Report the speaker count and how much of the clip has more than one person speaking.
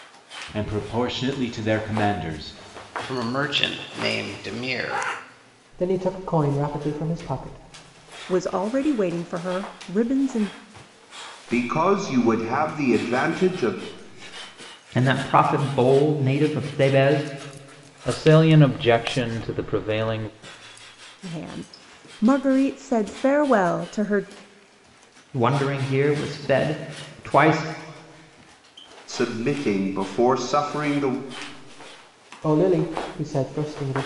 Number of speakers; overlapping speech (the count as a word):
seven, no overlap